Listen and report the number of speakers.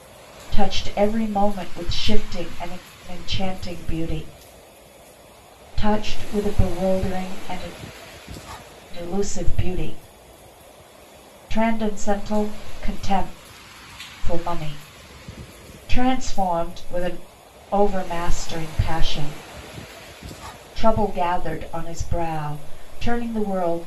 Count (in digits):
1